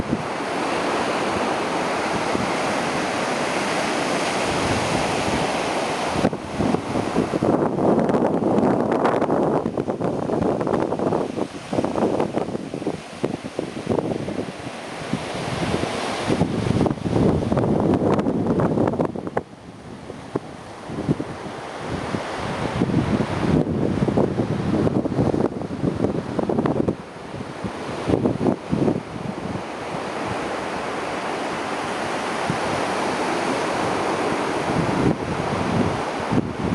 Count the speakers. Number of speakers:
zero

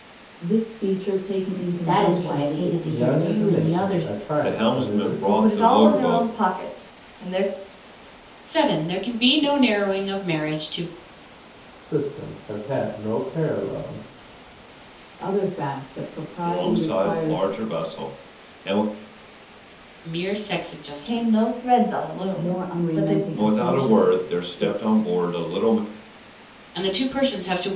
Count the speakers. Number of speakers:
six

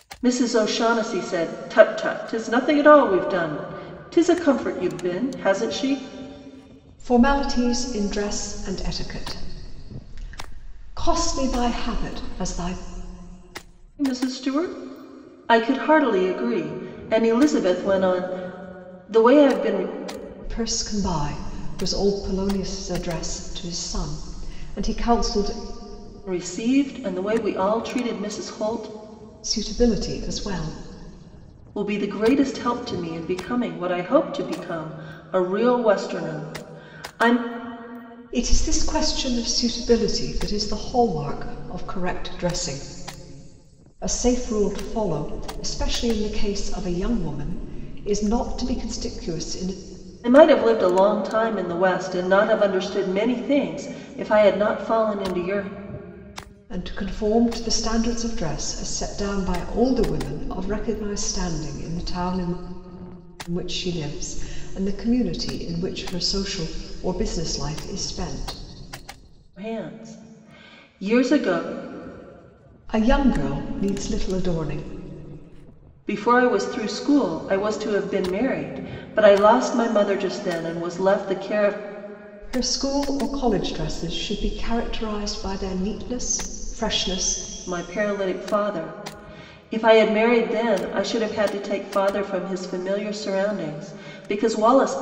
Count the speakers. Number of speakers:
two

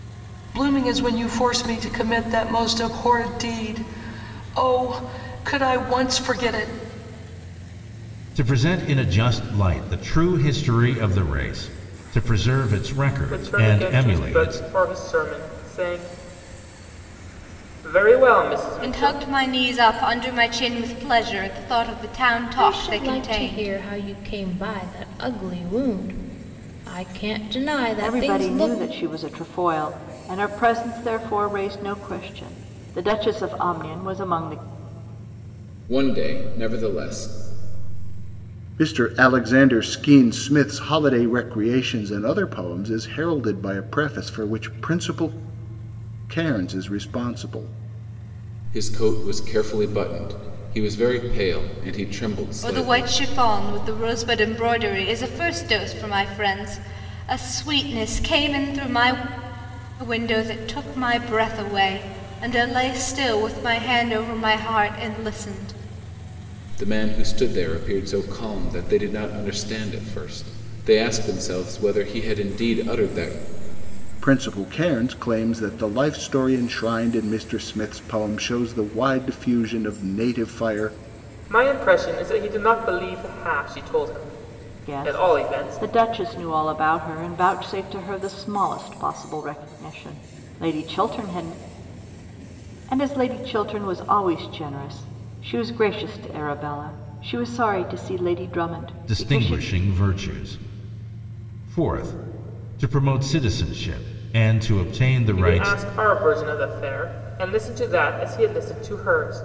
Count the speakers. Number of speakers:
eight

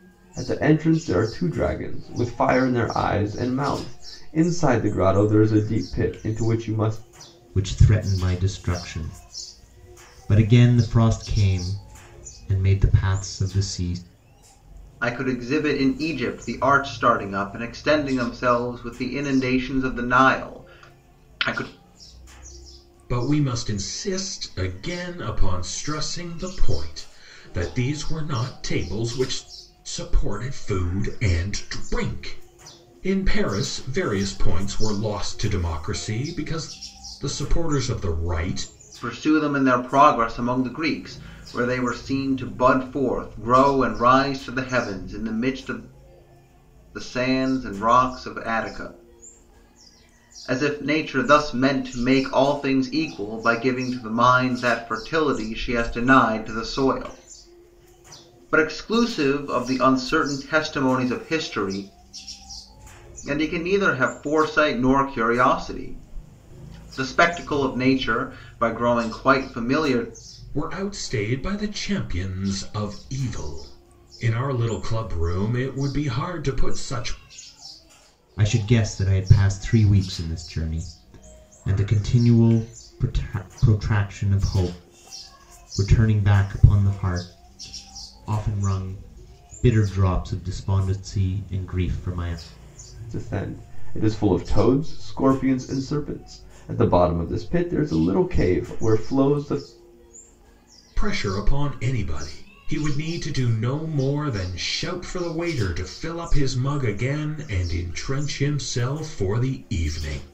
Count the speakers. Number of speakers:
four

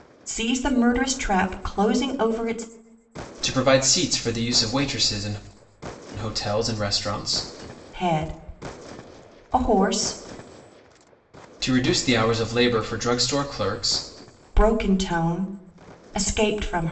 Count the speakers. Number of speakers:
two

